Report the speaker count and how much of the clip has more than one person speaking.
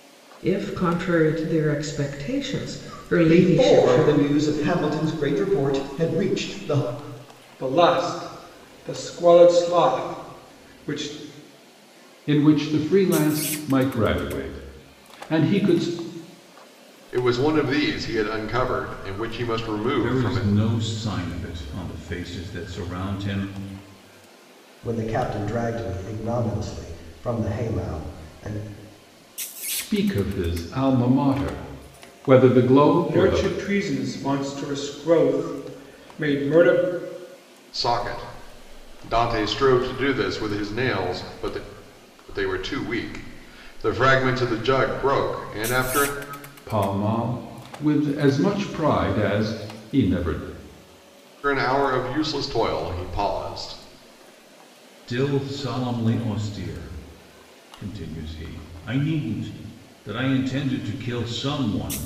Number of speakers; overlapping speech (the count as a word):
seven, about 4%